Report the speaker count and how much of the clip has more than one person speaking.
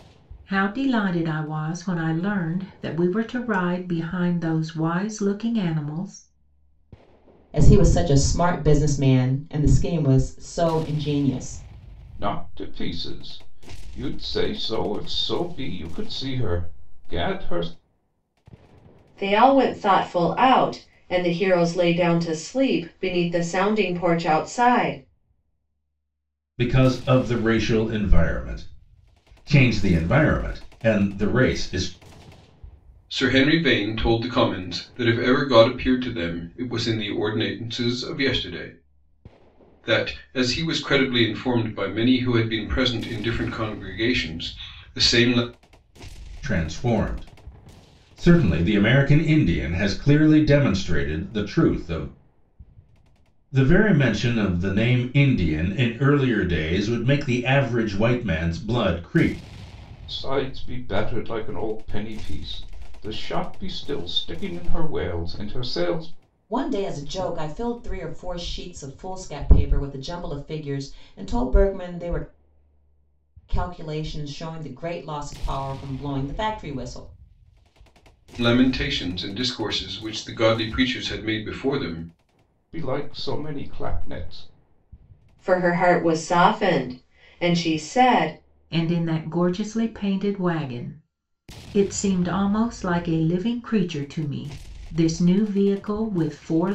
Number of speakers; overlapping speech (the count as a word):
six, no overlap